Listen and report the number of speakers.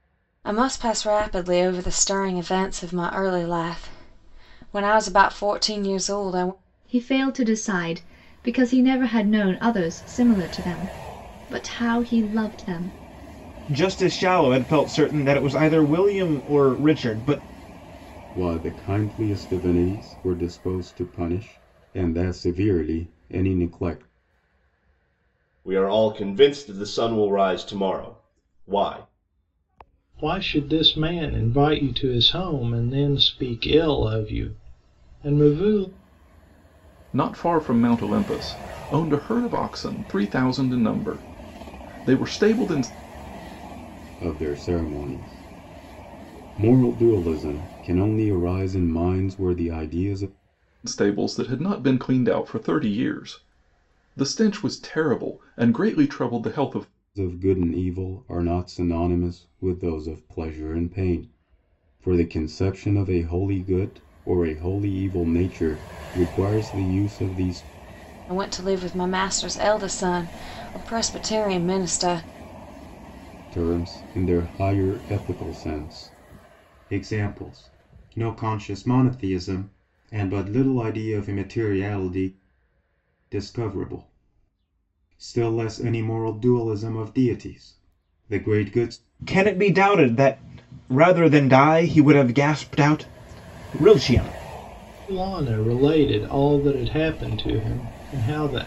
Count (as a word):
seven